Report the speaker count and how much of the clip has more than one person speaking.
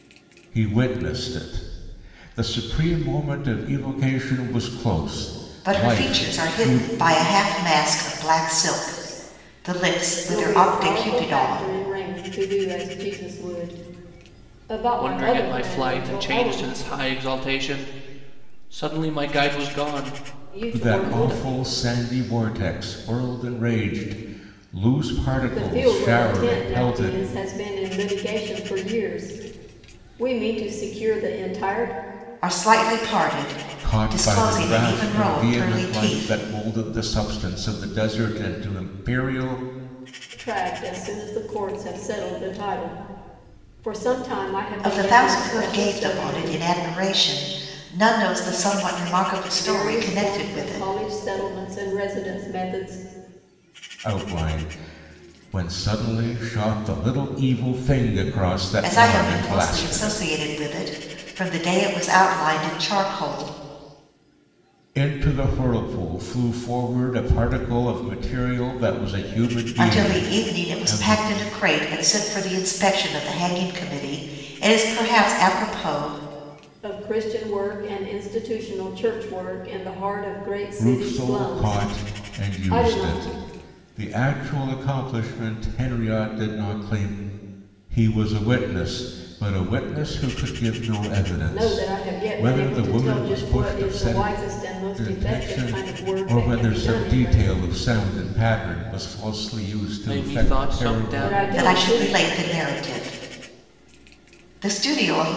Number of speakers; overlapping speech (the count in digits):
4, about 25%